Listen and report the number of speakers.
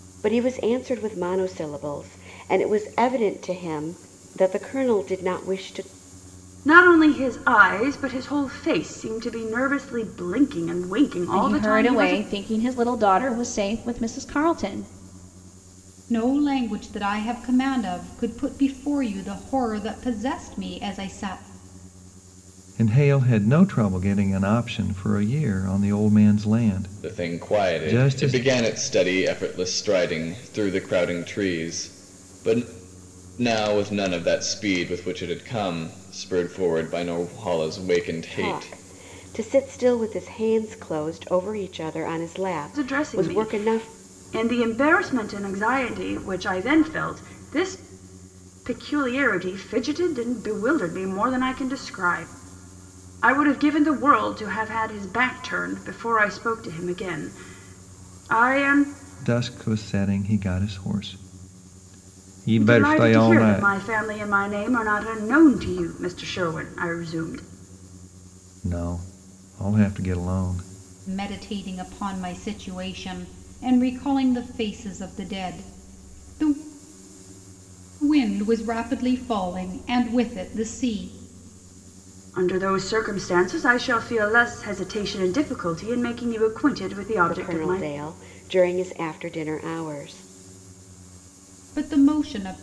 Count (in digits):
6